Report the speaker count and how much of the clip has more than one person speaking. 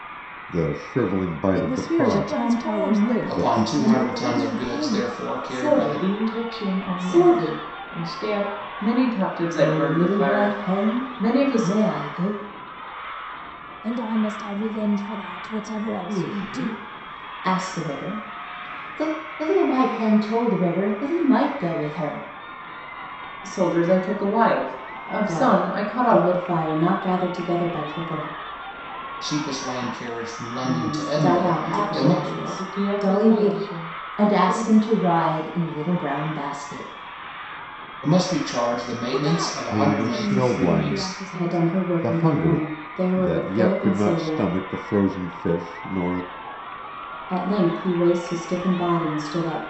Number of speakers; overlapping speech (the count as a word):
eight, about 36%